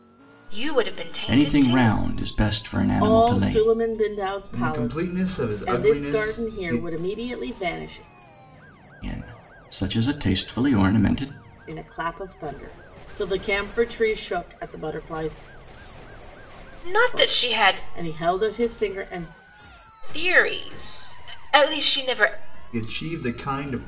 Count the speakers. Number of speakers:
four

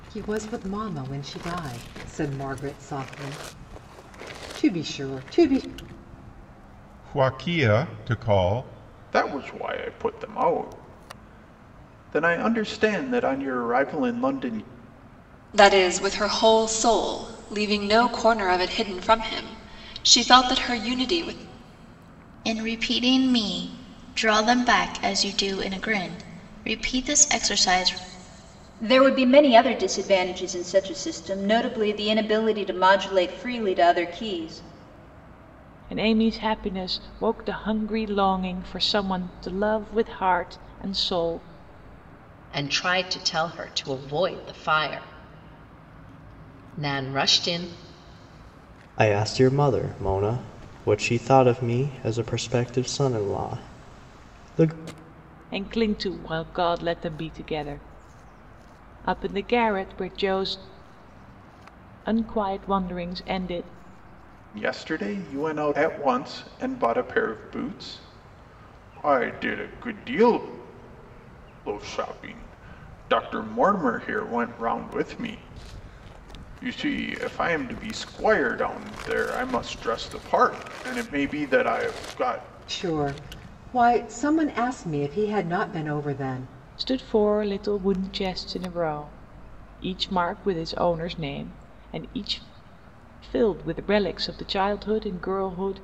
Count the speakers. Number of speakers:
nine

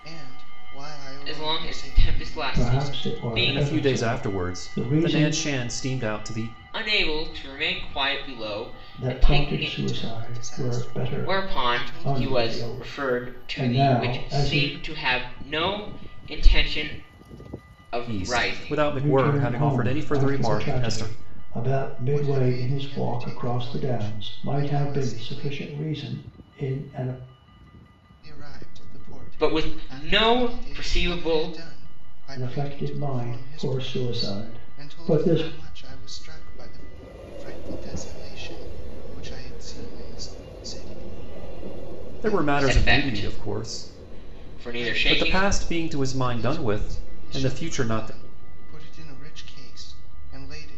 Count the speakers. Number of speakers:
four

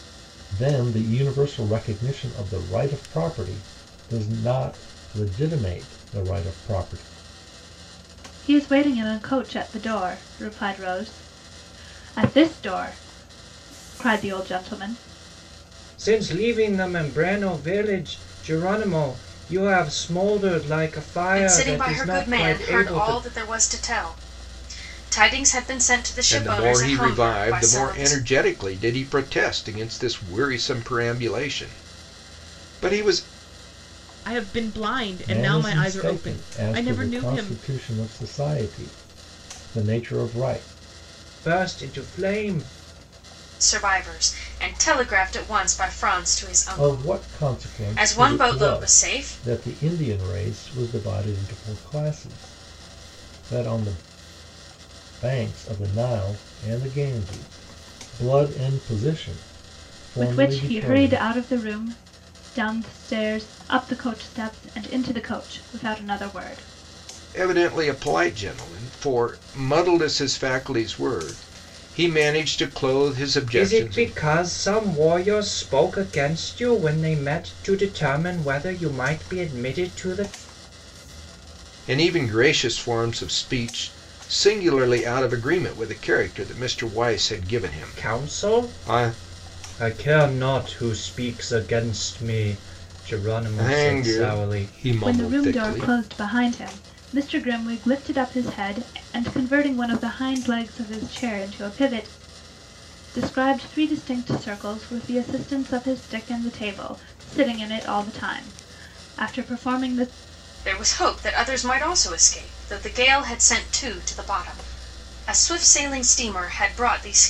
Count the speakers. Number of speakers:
six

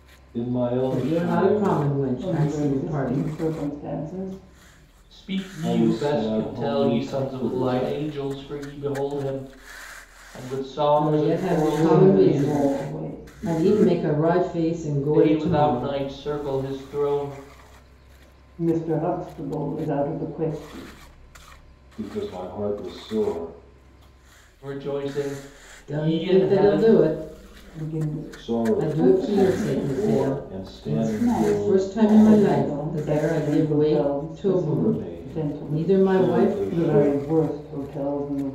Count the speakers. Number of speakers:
four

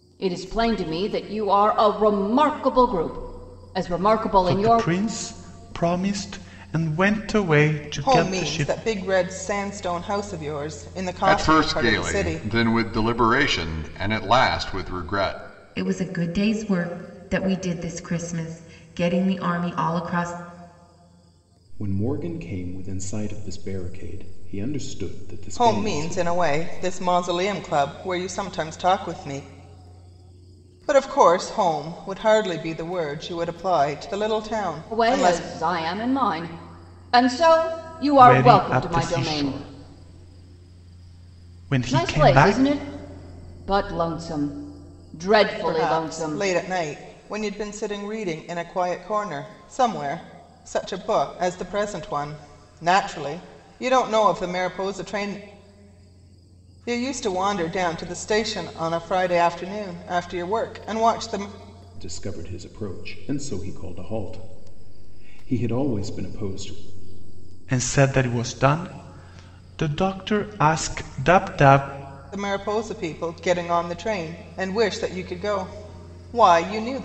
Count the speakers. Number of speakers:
six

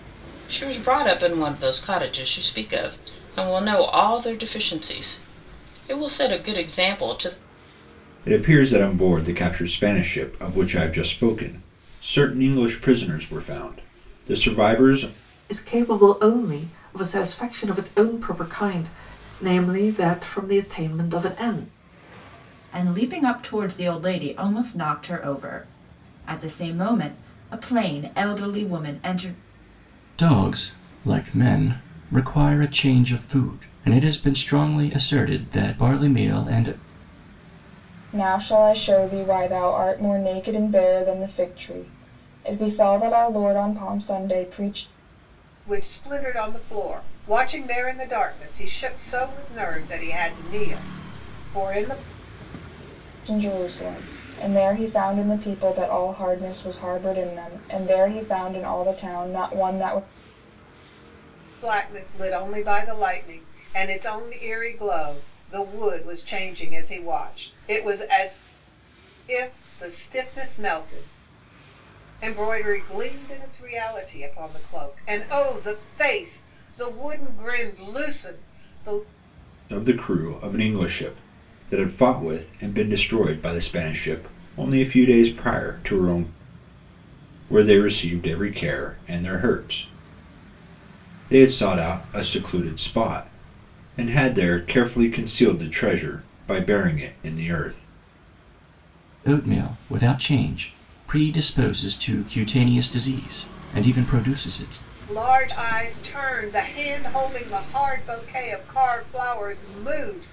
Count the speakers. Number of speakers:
seven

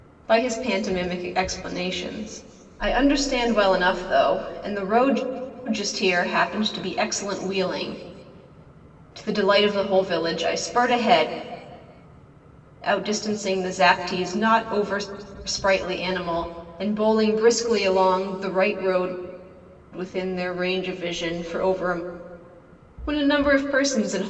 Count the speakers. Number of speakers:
one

